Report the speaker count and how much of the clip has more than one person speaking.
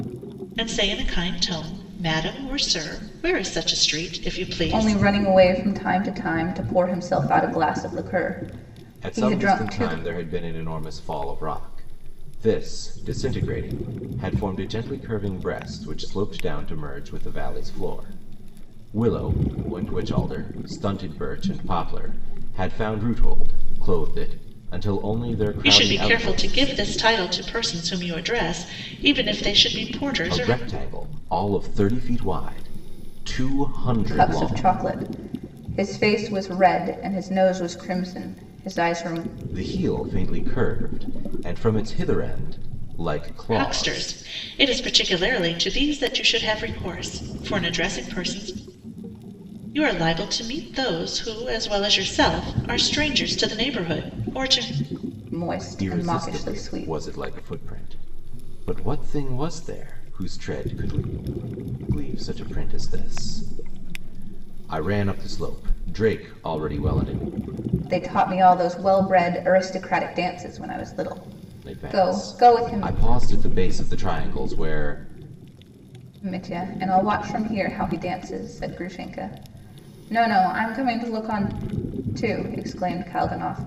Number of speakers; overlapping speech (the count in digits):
3, about 8%